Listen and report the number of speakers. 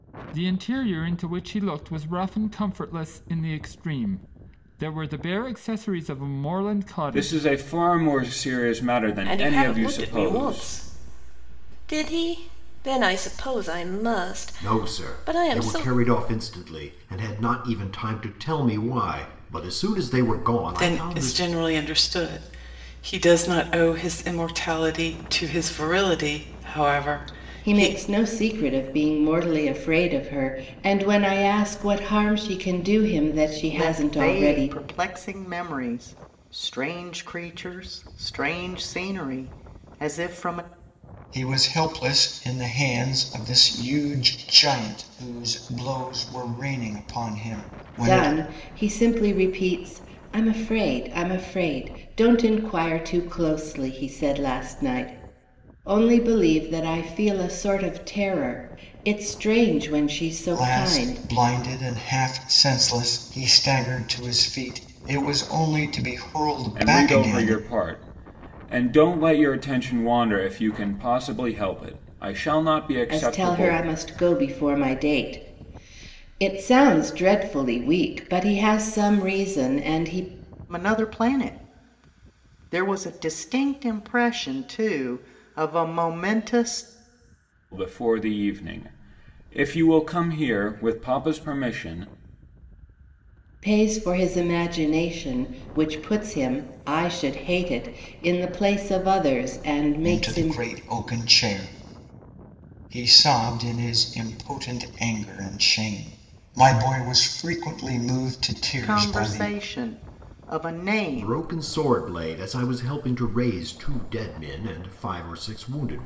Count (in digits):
8